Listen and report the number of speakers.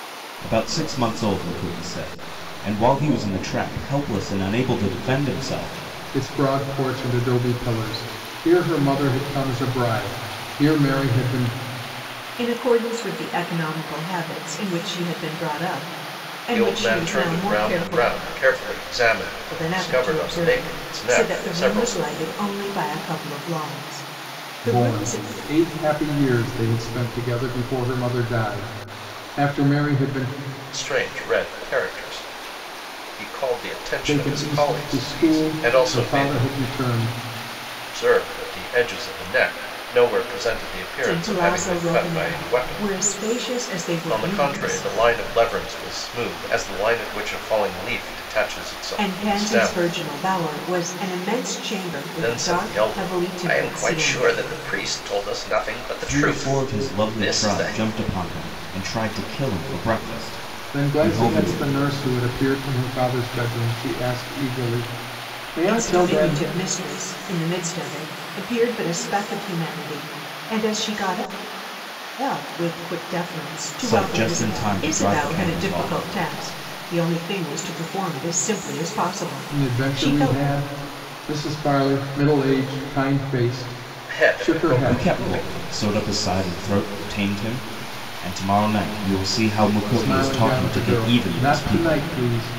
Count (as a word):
four